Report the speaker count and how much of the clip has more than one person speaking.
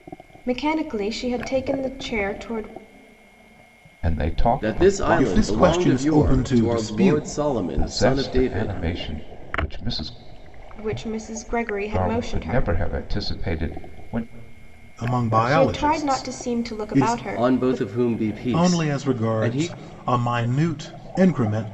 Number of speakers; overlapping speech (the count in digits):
4, about 38%